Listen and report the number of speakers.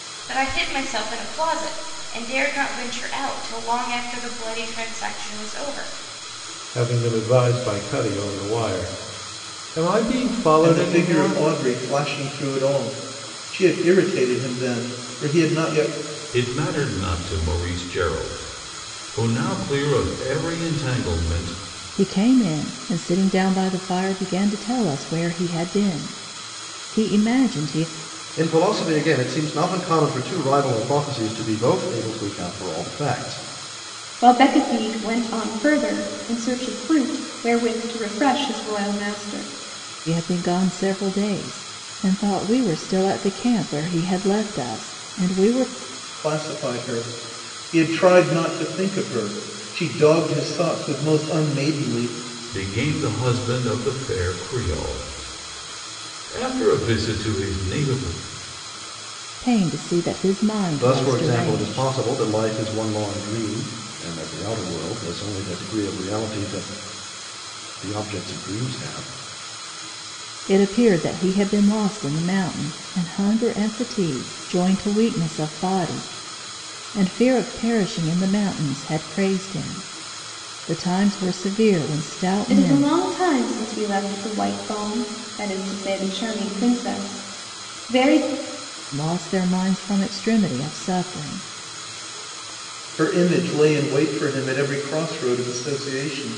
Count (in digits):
7